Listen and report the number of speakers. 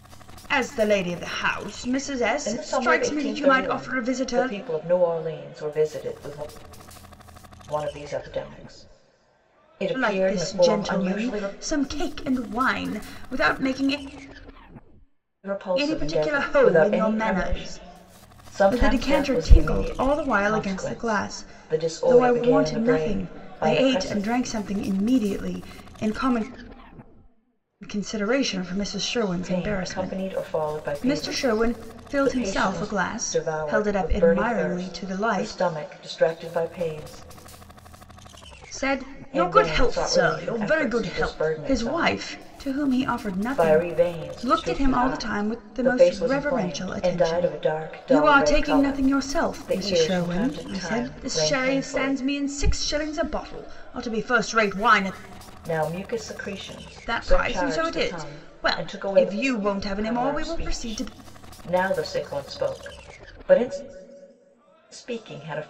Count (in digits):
2